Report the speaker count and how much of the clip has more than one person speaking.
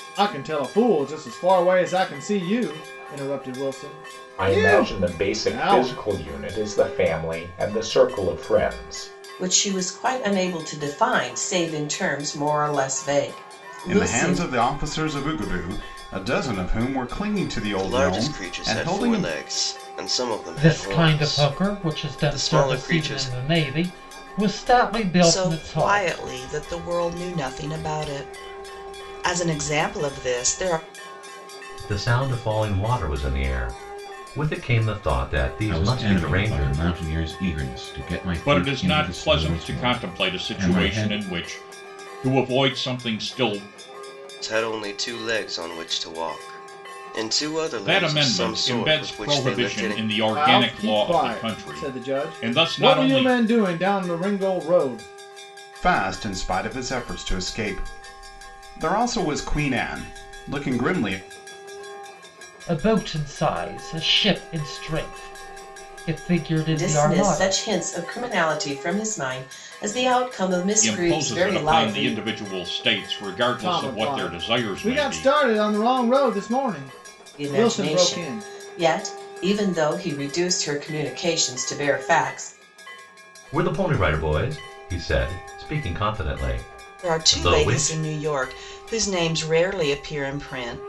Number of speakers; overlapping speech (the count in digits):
10, about 25%